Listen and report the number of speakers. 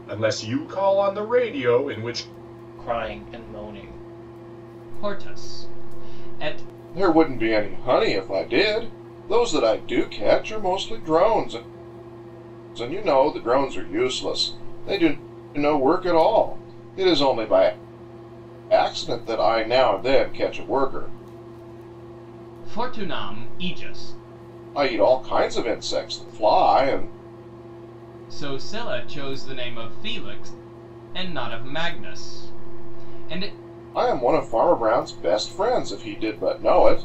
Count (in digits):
4